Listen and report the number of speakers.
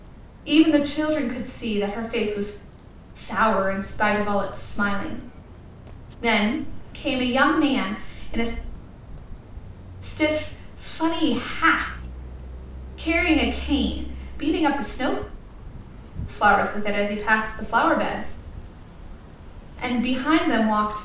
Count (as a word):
one